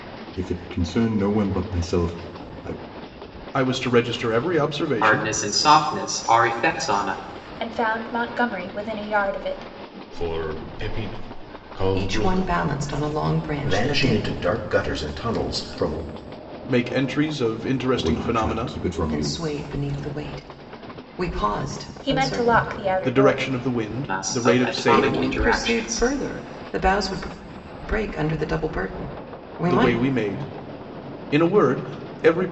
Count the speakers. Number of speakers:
seven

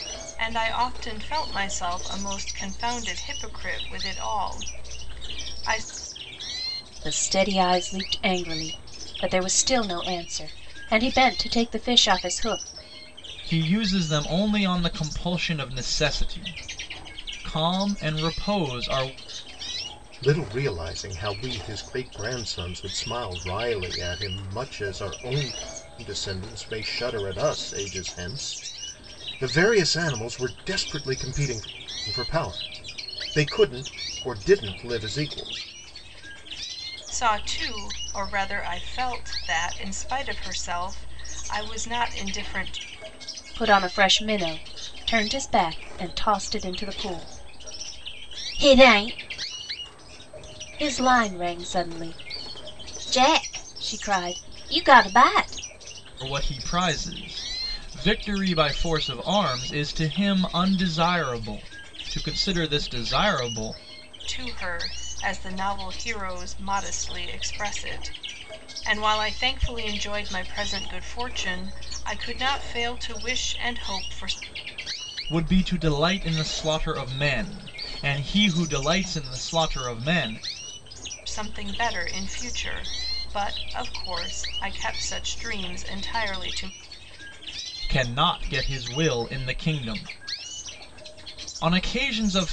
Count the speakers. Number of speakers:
four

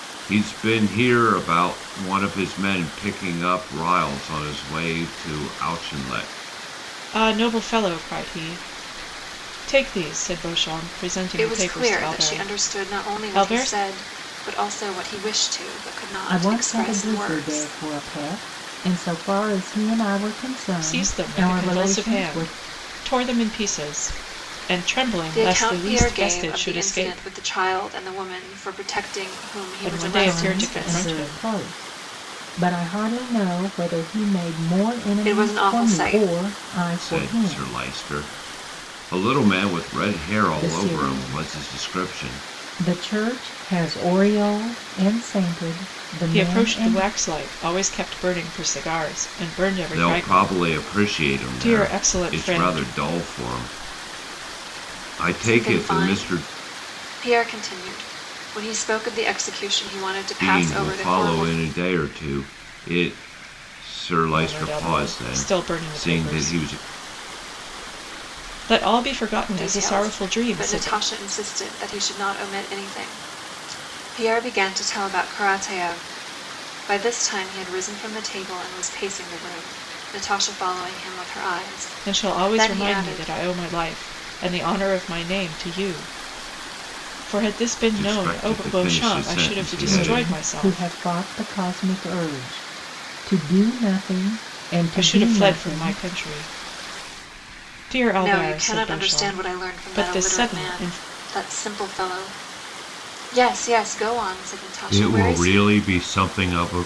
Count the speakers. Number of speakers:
four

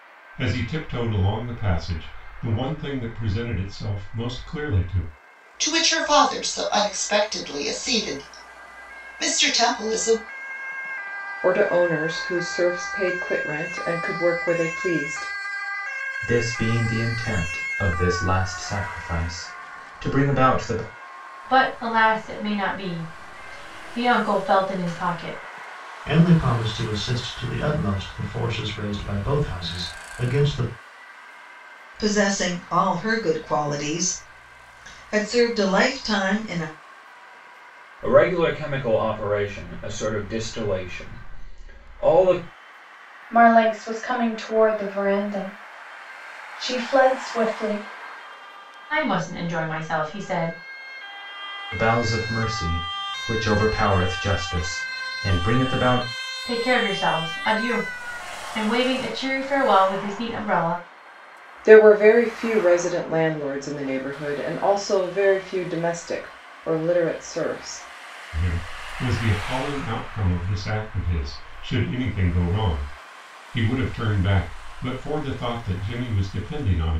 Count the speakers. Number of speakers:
nine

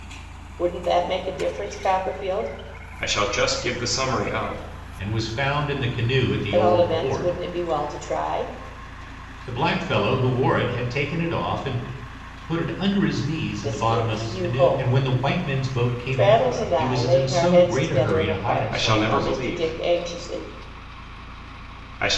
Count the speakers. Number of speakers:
three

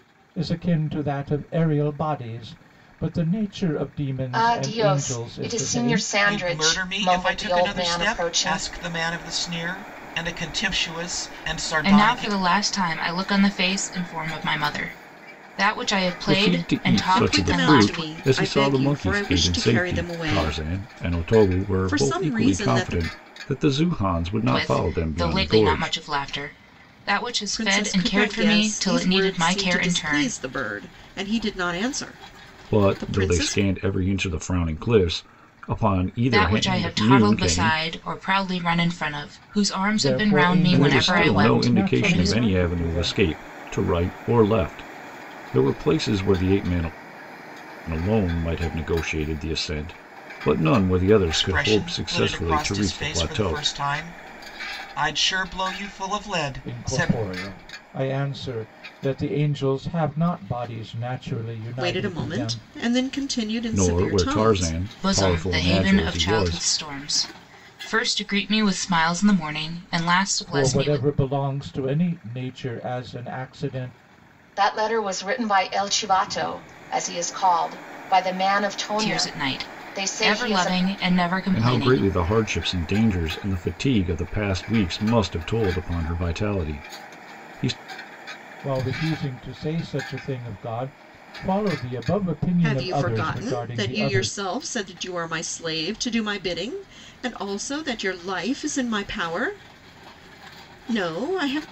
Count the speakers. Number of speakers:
six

